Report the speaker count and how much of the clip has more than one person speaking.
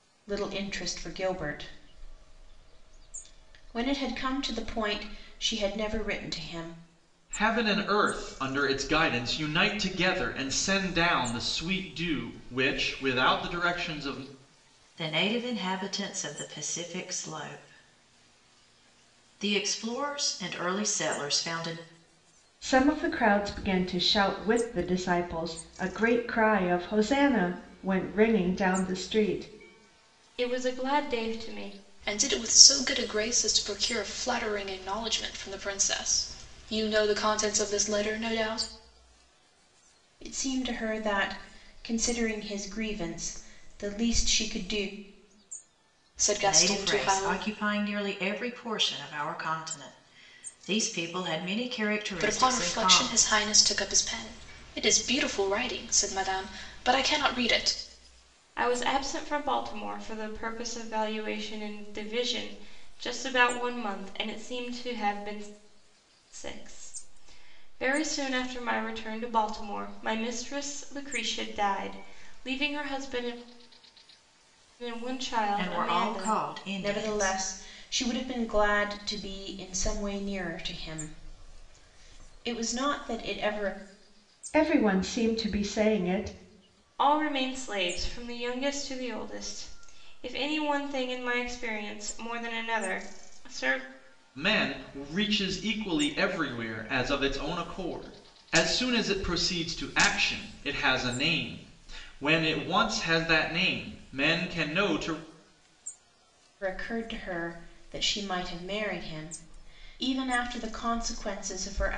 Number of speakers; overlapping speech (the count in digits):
6, about 3%